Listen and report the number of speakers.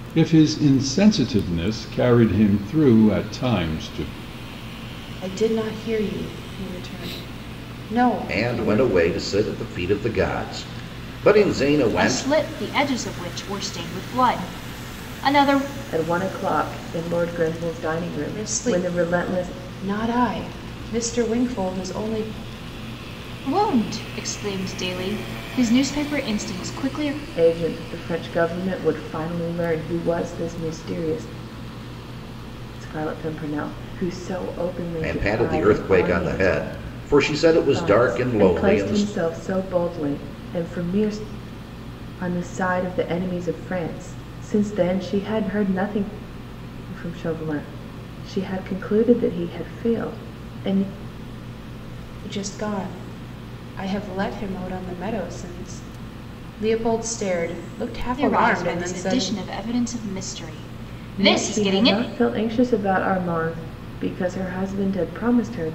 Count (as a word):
five